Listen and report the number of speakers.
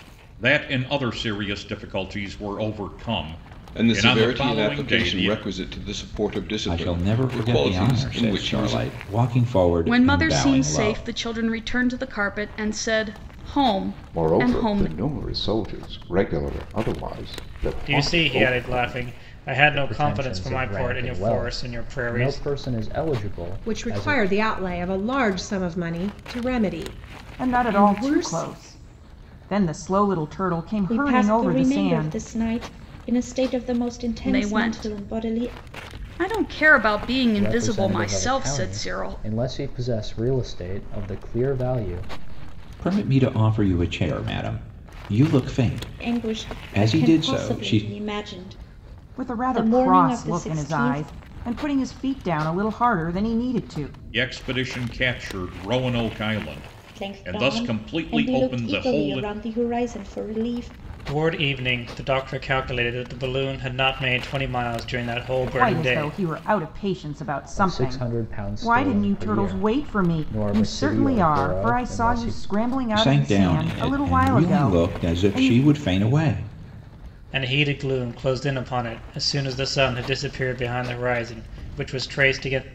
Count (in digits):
10